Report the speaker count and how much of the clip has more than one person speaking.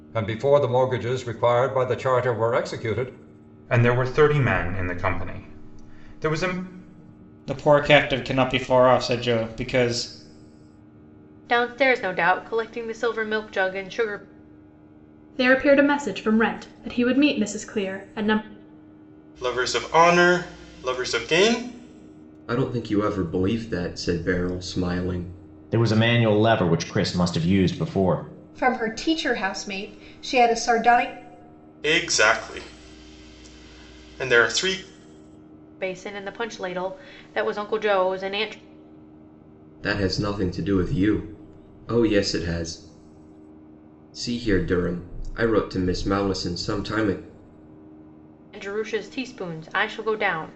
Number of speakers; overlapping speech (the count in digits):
9, no overlap